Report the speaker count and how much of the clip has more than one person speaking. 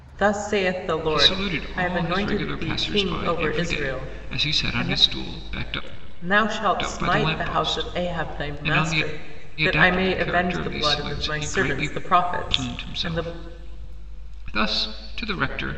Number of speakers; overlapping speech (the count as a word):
two, about 60%